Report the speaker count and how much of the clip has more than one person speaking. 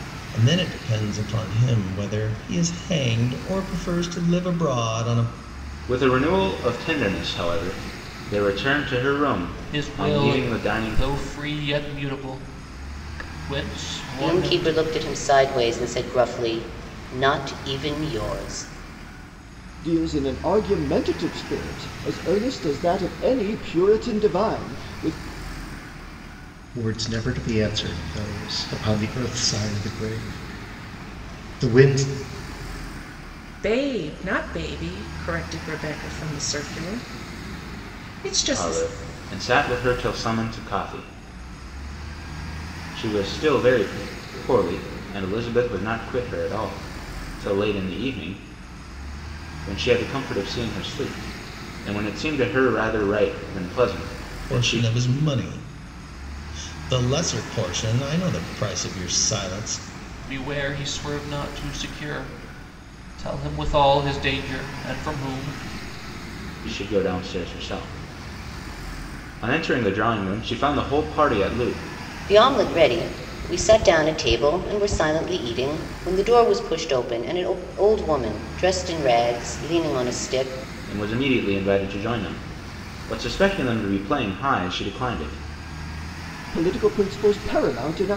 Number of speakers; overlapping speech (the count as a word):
seven, about 3%